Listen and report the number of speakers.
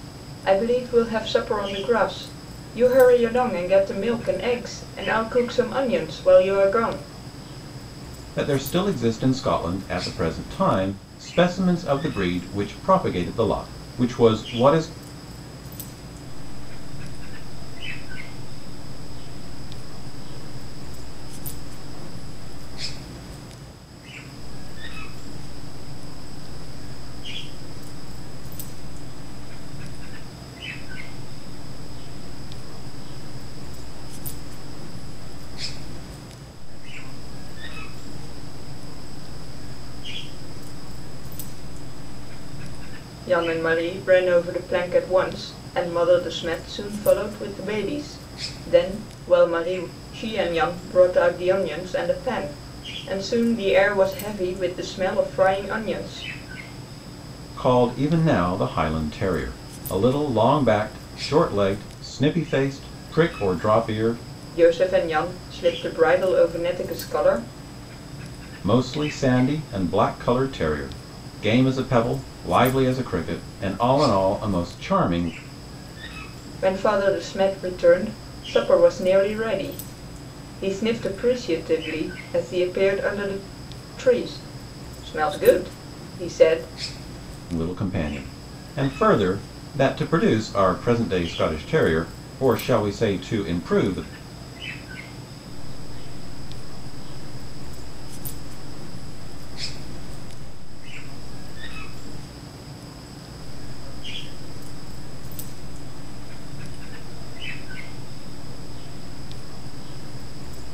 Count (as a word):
three